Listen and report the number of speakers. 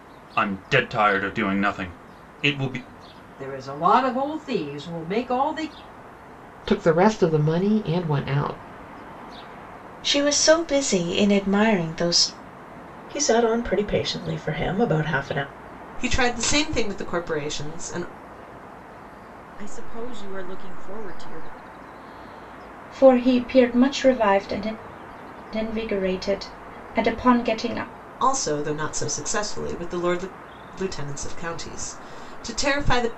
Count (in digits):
8